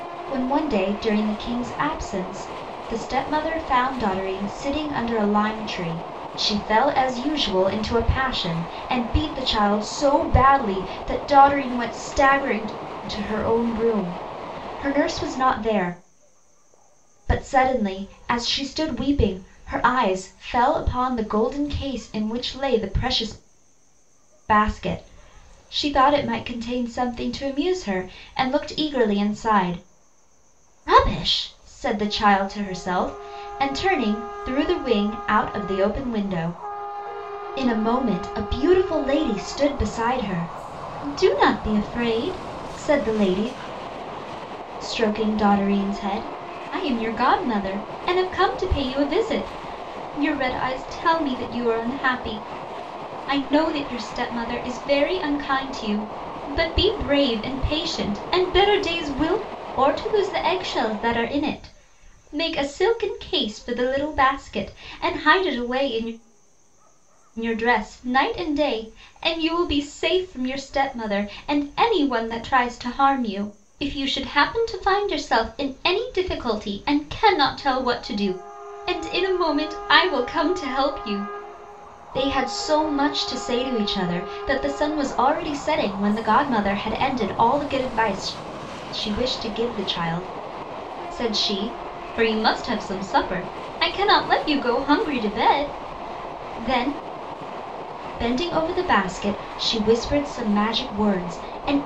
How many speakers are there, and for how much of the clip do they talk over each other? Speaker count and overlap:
one, no overlap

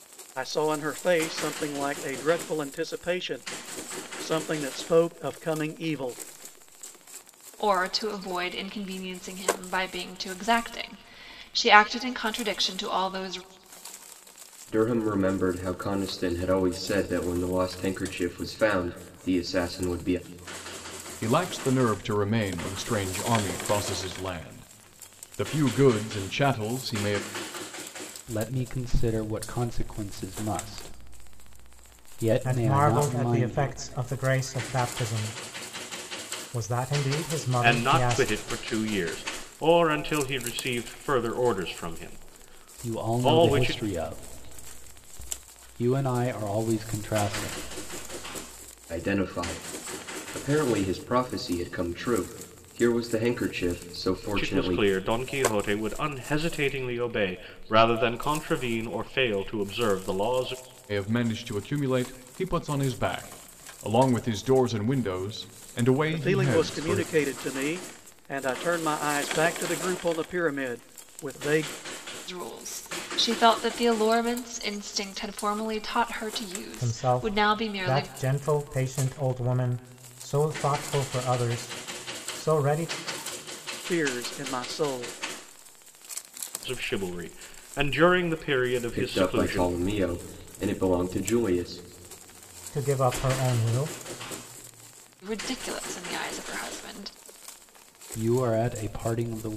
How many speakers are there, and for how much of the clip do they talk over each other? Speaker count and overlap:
seven, about 7%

